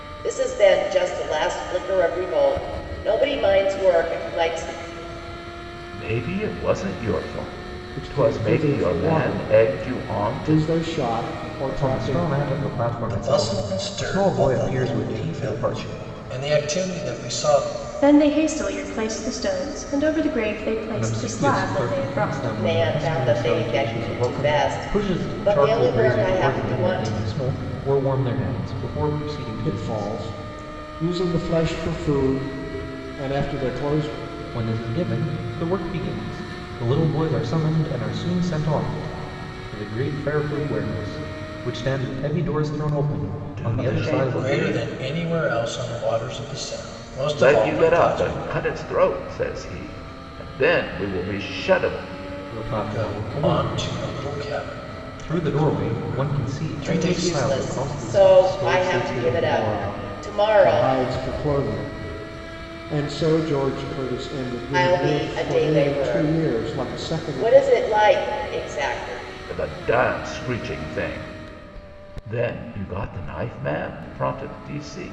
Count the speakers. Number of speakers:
six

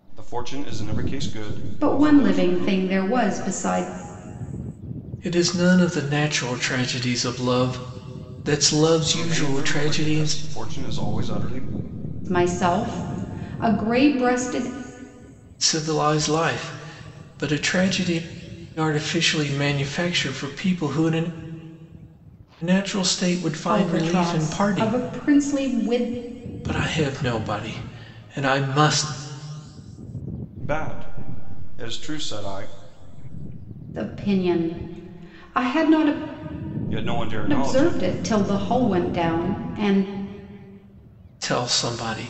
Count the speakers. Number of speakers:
three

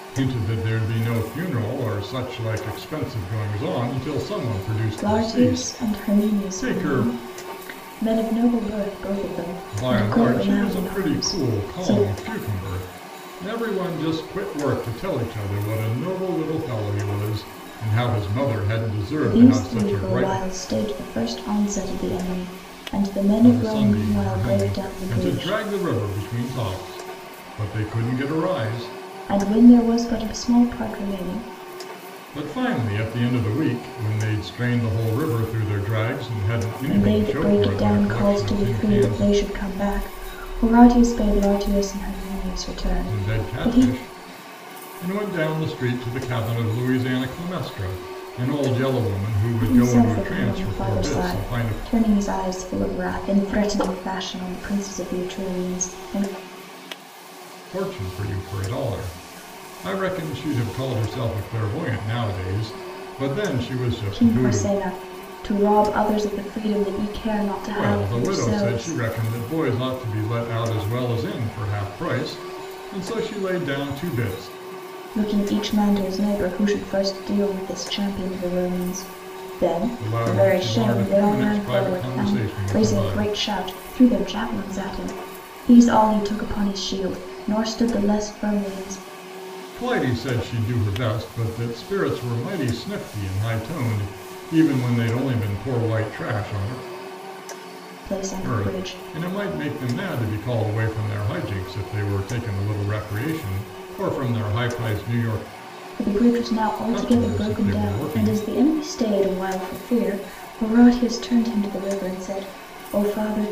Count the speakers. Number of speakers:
two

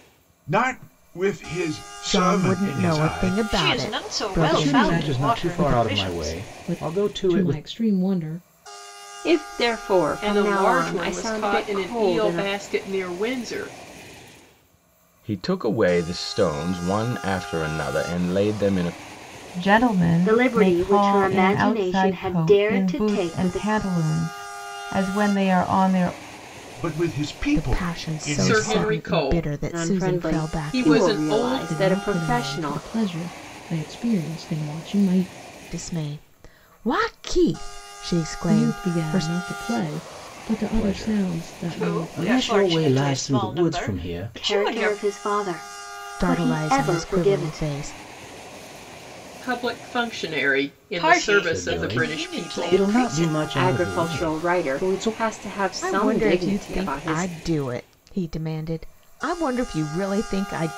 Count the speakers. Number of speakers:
ten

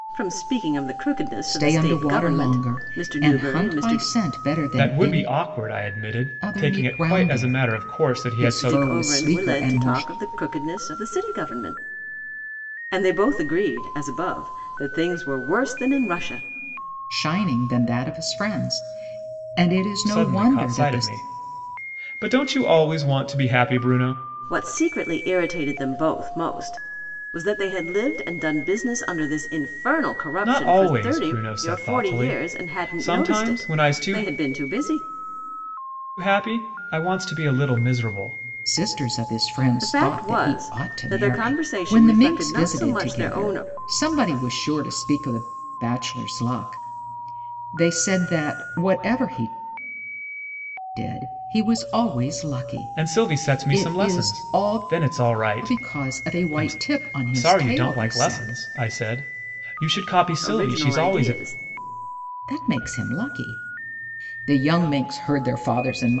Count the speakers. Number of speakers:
three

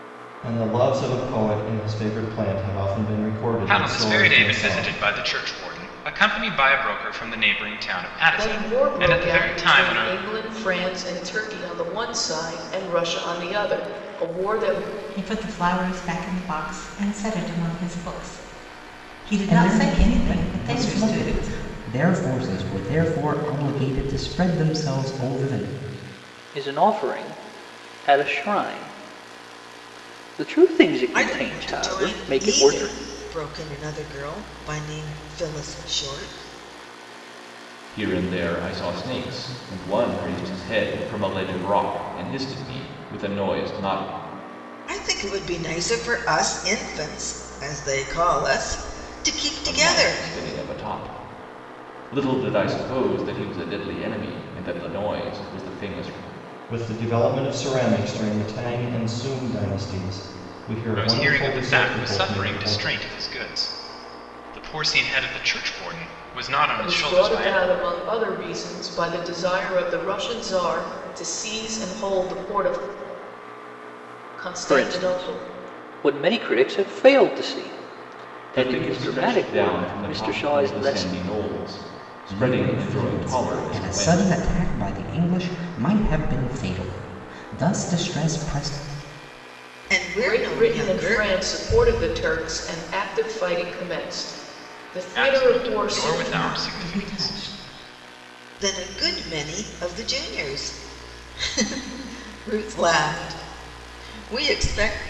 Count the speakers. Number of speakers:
eight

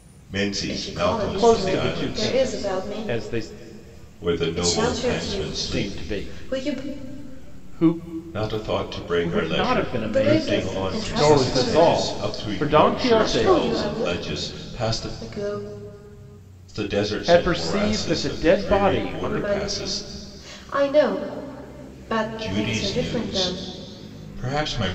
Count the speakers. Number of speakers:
three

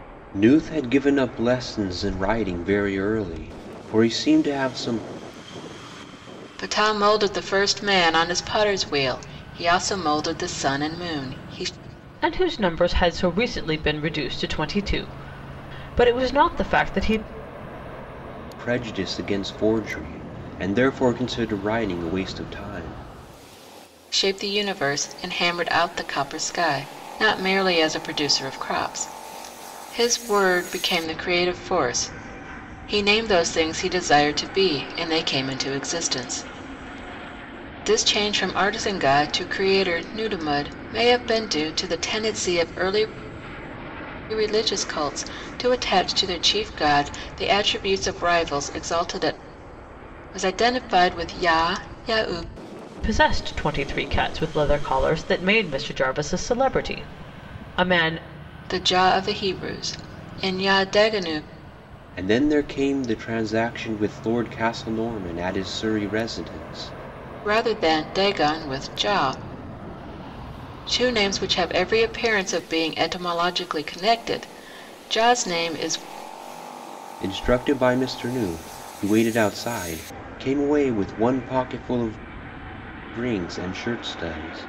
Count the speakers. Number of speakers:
three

